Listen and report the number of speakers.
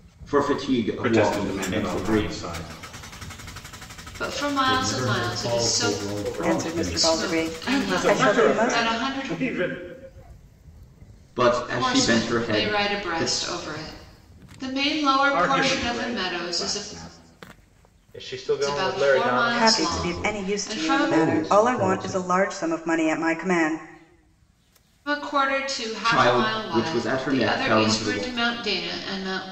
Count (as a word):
six